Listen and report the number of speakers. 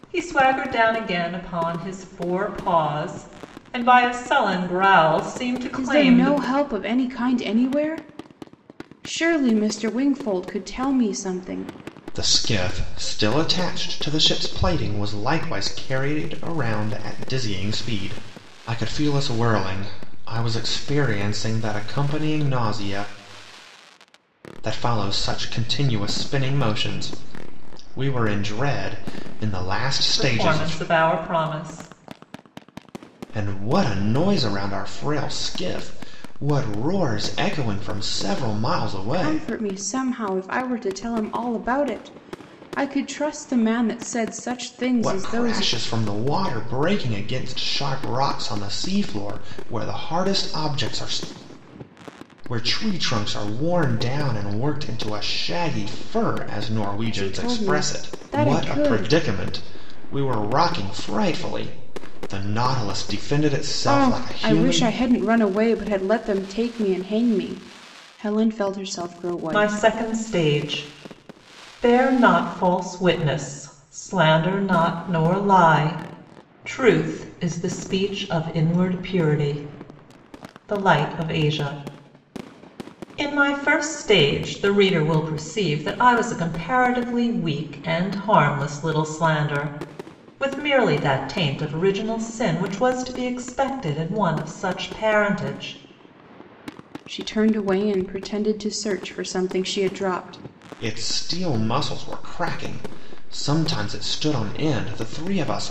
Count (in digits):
3